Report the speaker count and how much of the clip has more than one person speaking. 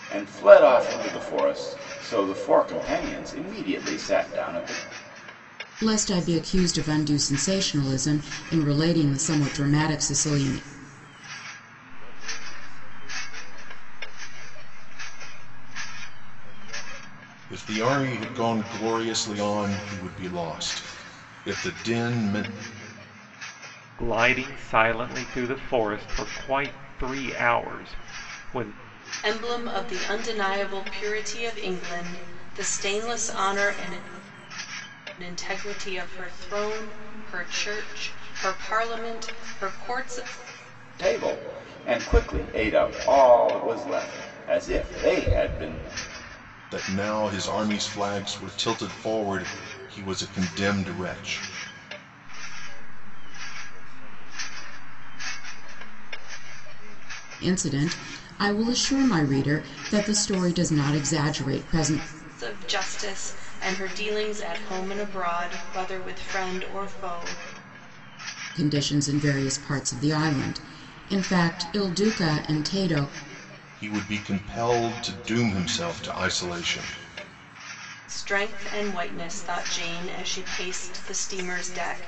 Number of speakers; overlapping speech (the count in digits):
6, no overlap